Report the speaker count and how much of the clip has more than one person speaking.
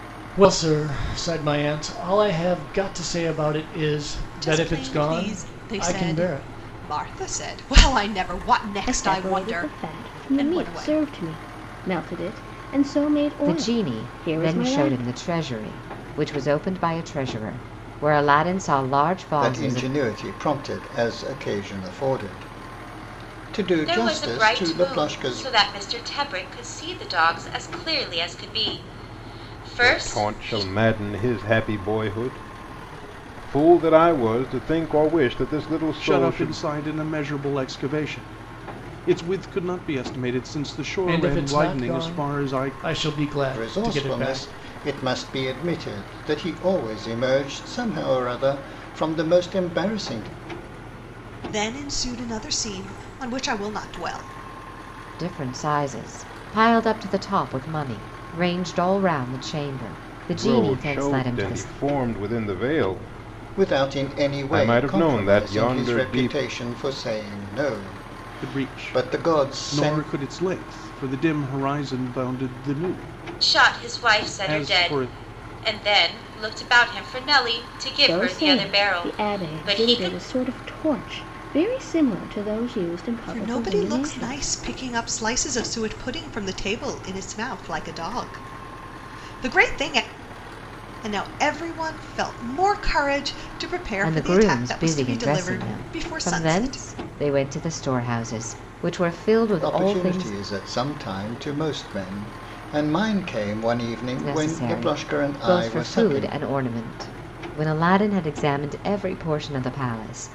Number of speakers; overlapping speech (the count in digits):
8, about 27%